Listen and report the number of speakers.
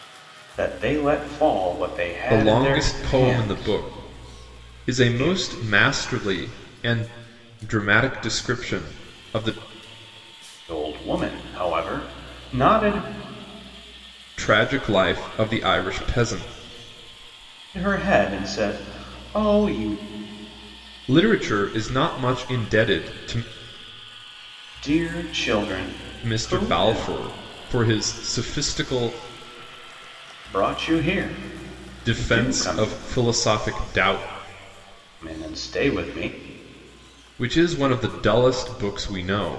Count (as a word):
two